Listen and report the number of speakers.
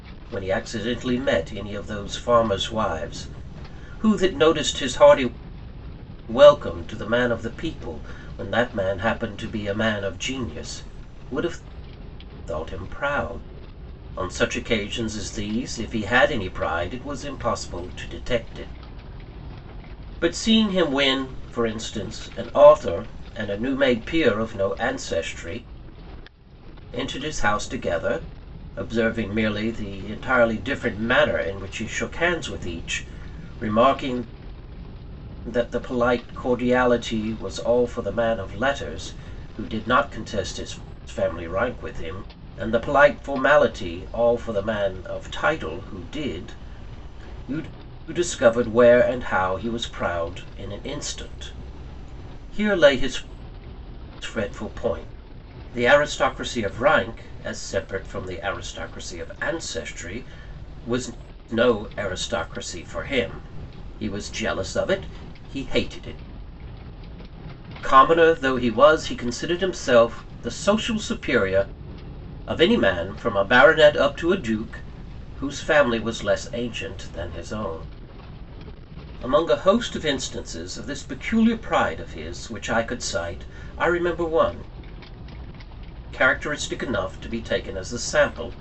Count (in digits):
1